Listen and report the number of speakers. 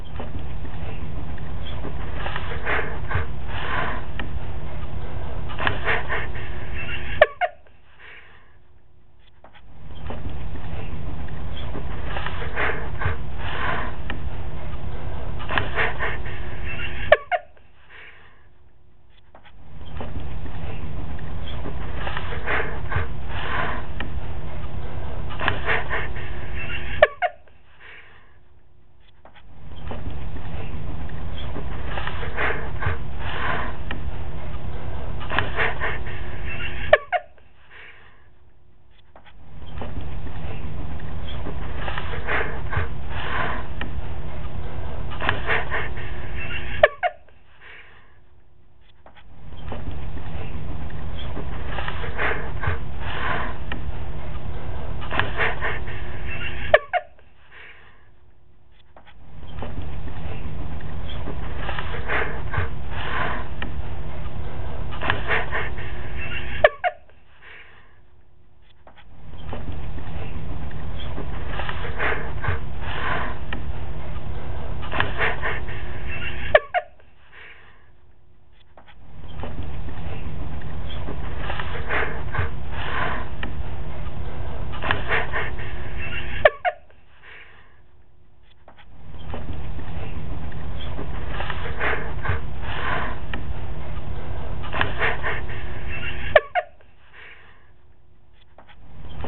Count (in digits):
0